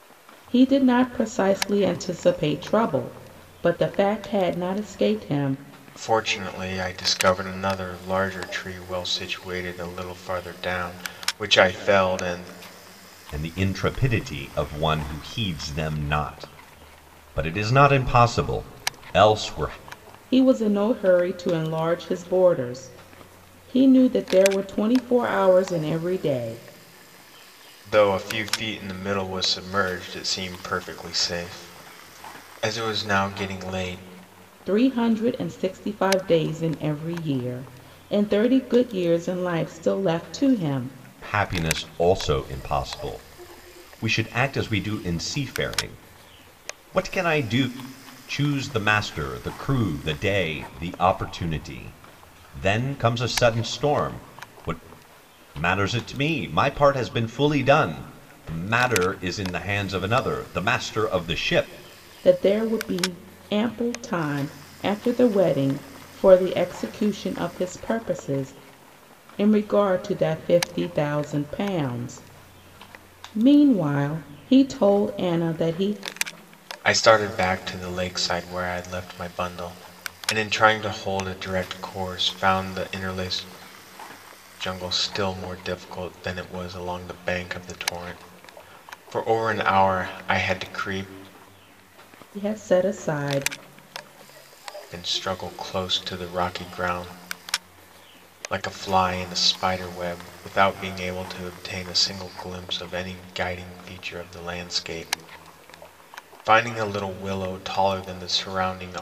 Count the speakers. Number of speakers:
3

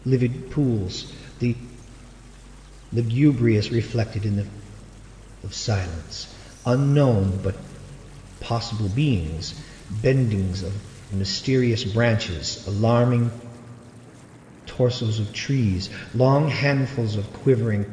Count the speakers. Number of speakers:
1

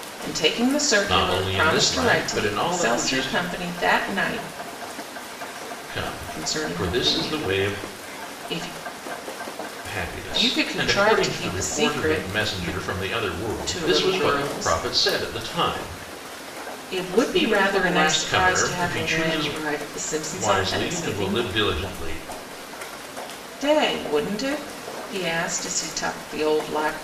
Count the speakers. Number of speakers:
2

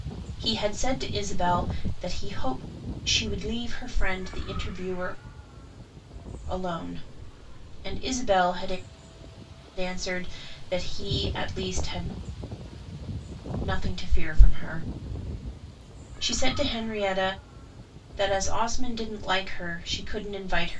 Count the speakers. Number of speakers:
1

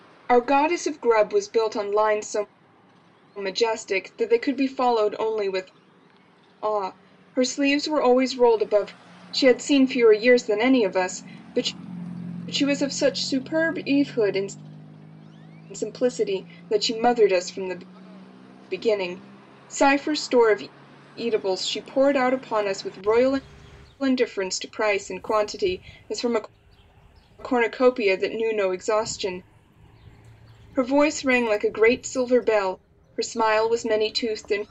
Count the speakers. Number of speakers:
1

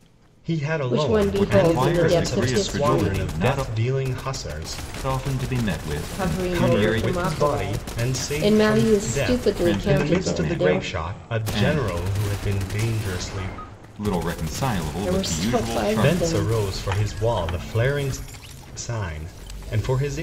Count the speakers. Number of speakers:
3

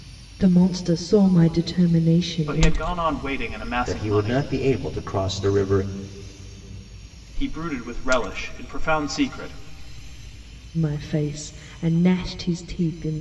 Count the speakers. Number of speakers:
3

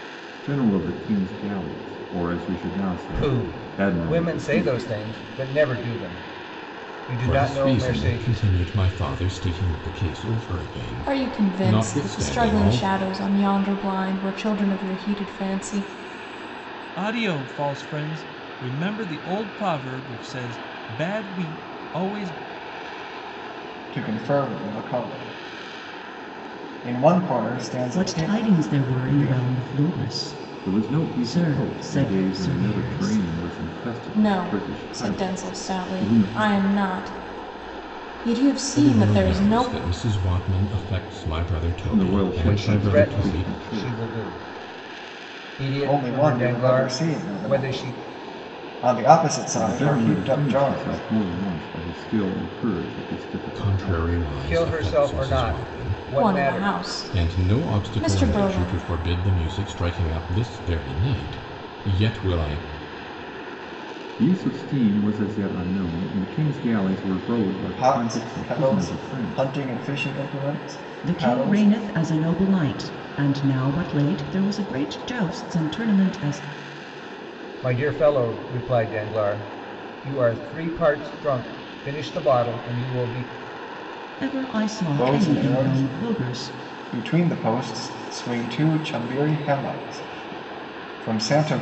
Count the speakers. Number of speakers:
7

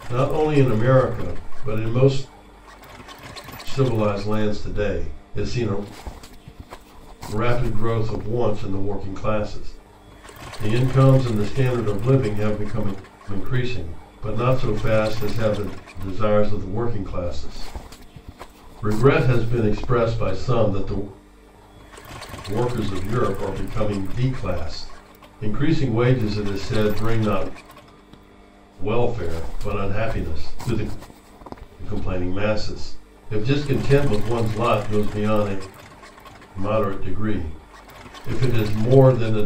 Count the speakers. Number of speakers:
1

